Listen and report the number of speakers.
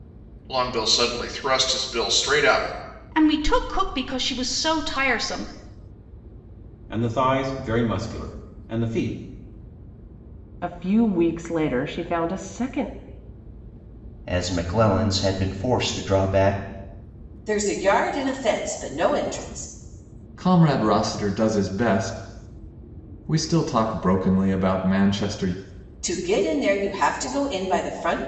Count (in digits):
7